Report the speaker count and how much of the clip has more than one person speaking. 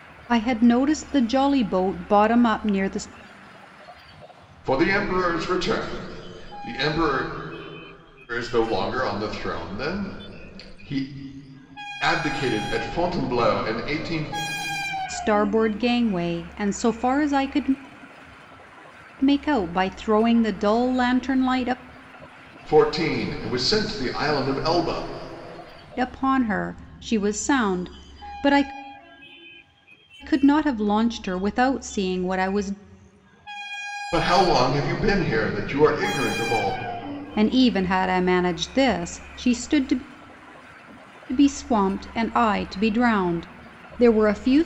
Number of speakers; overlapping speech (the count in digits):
2, no overlap